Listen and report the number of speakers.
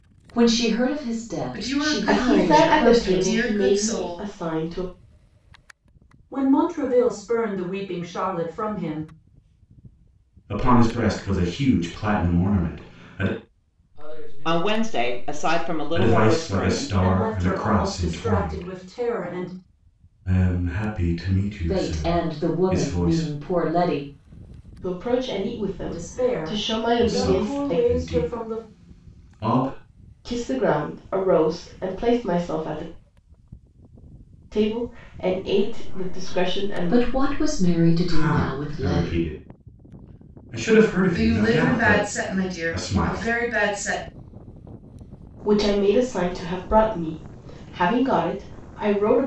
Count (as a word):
seven